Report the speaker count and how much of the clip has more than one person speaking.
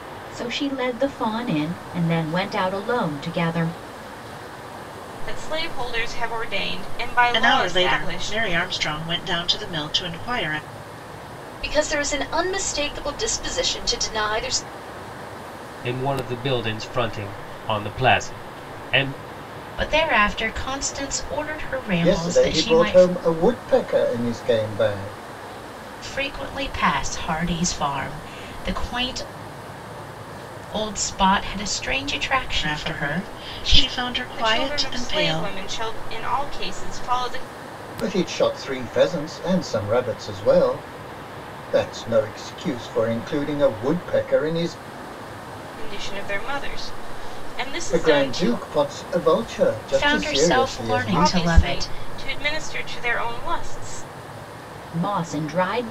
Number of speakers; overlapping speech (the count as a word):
seven, about 14%